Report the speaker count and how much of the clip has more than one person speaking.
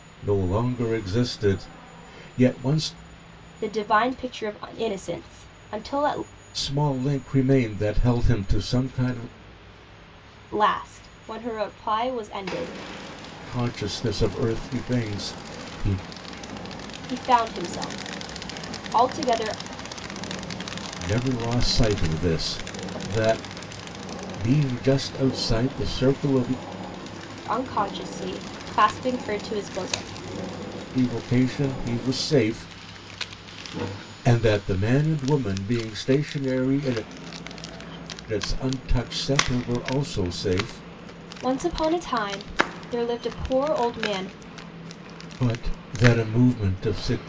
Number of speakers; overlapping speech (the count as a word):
two, no overlap